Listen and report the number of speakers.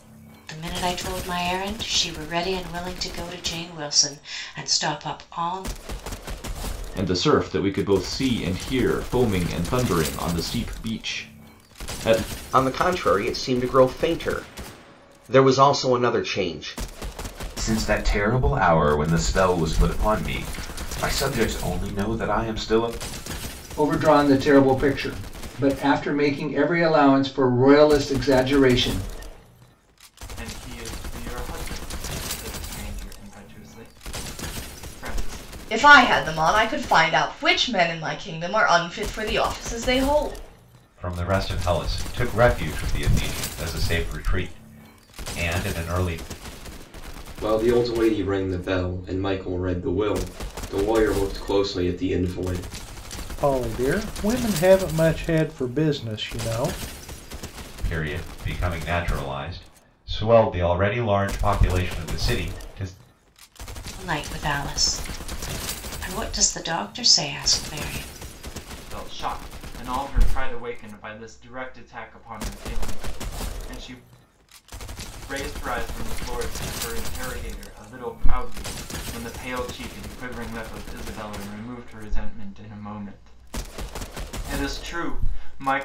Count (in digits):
10